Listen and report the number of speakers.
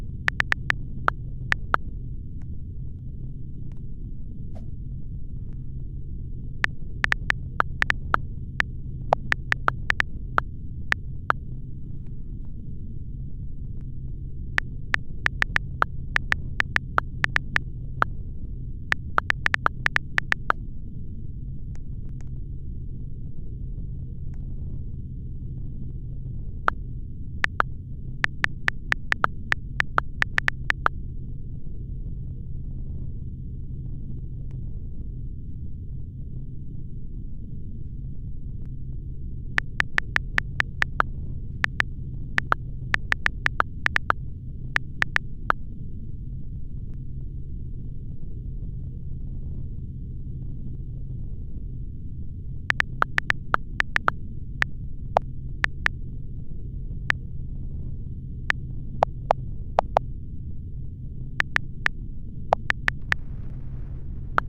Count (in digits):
0